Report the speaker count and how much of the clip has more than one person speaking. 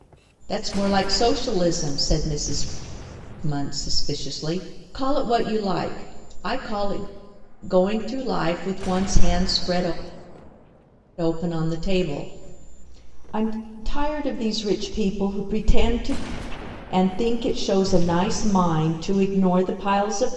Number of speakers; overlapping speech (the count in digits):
1, no overlap